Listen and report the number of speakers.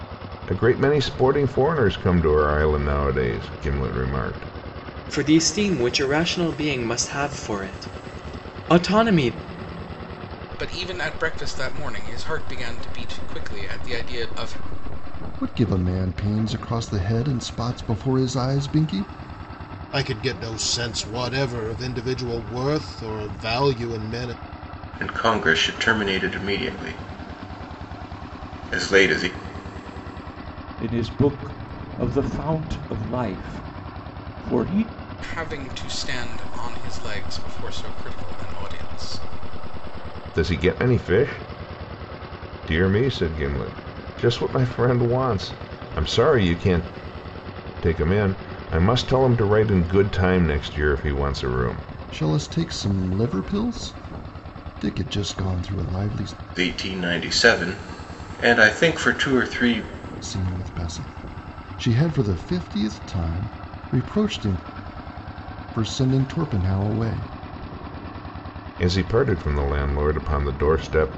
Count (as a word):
seven